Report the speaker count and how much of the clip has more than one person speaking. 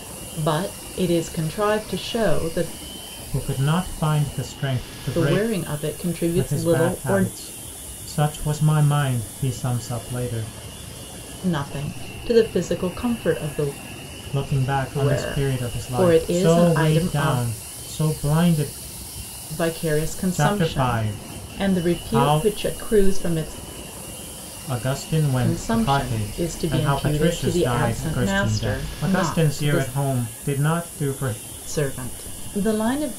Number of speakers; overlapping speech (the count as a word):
two, about 30%